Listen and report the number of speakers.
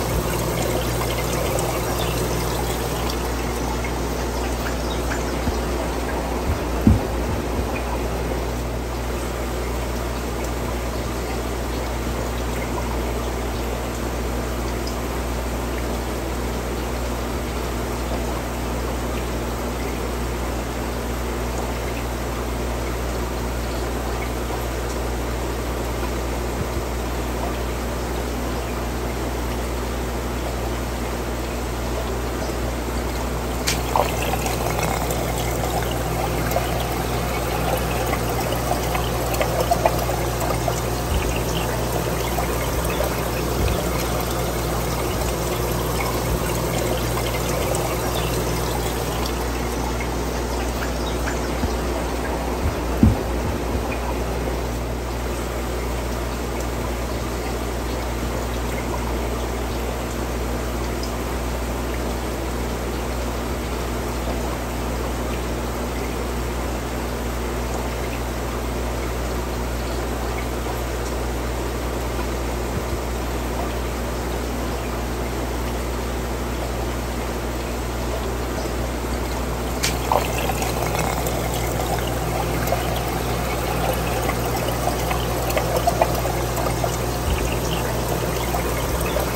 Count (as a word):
zero